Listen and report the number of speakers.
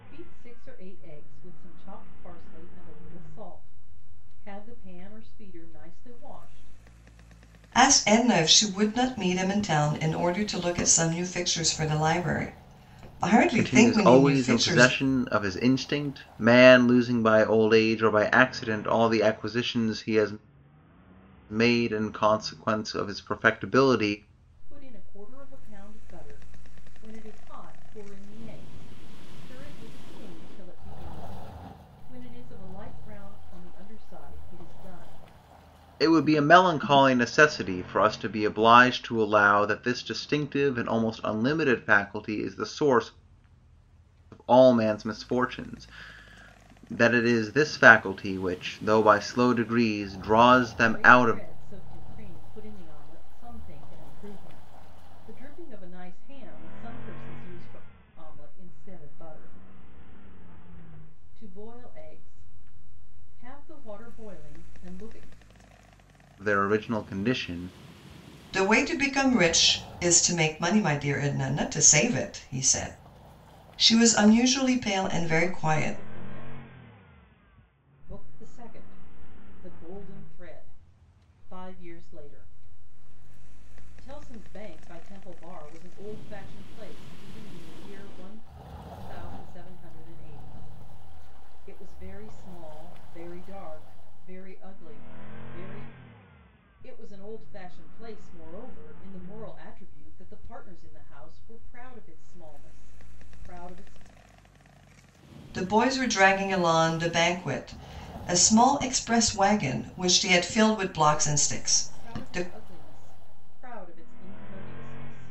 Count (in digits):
3